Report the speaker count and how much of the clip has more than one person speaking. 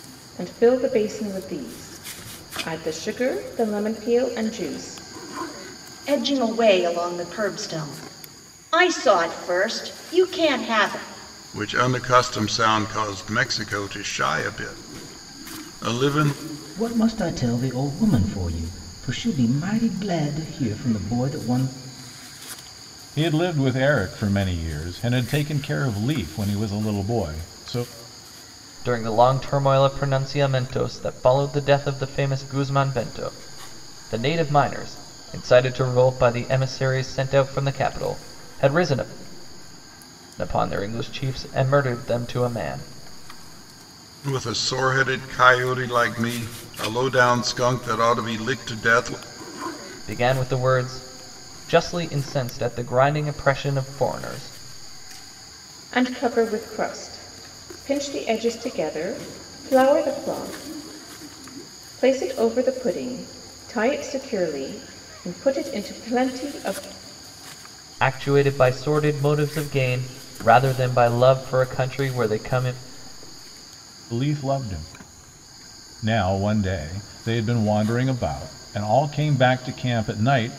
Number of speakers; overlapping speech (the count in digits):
6, no overlap